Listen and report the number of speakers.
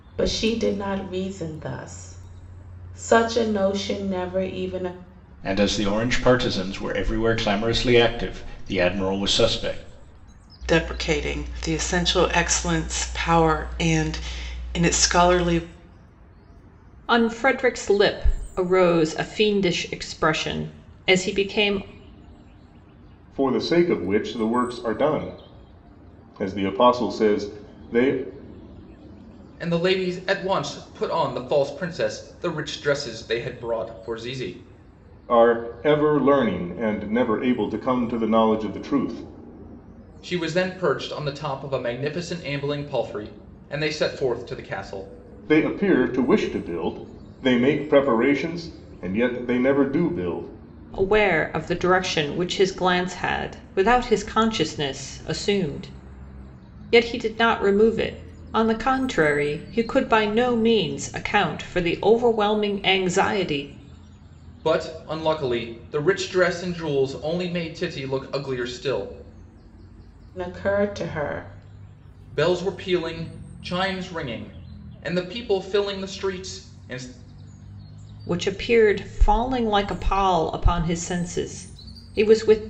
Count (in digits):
6